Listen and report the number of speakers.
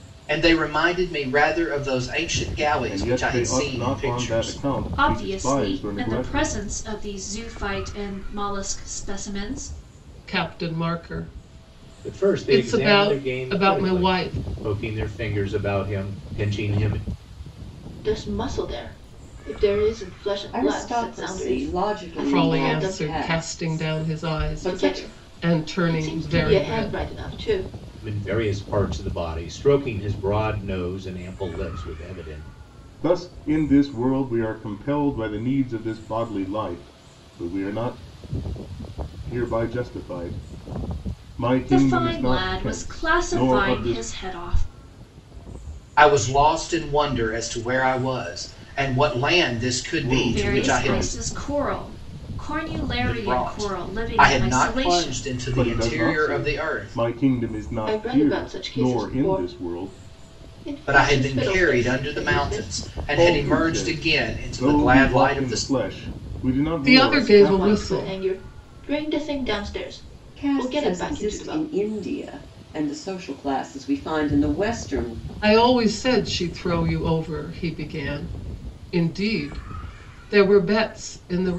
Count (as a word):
seven